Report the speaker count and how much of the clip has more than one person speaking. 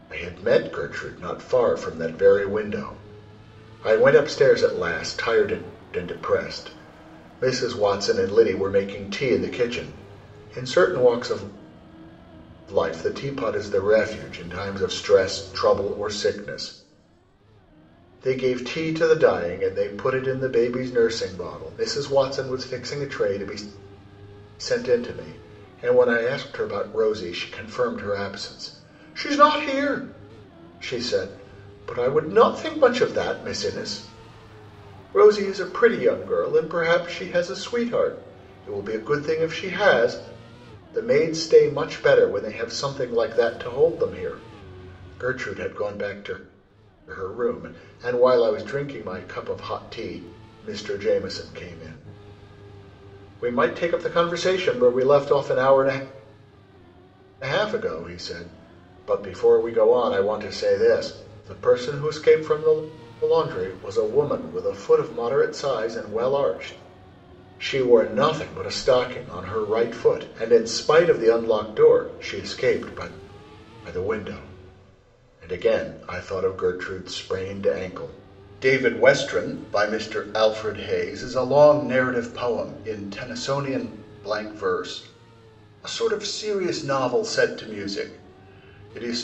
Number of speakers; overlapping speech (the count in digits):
1, no overlap